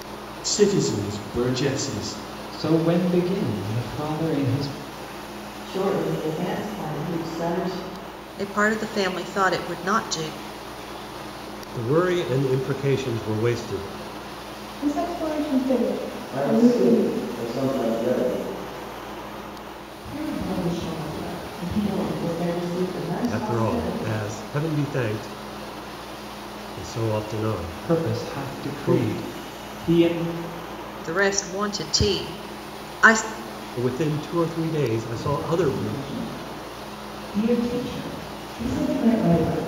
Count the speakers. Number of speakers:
8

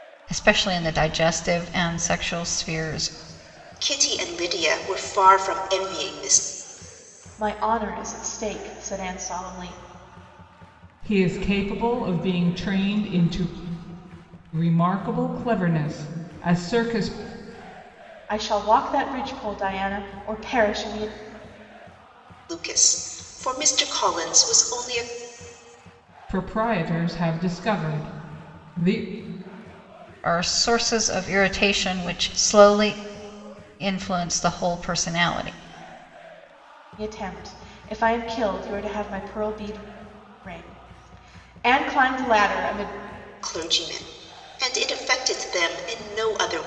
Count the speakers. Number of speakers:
4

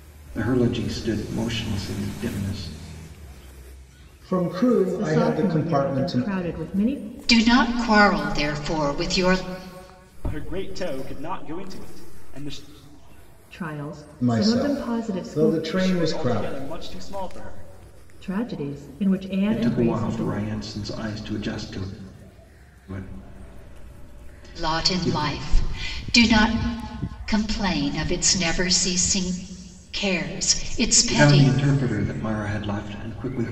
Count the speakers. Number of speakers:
5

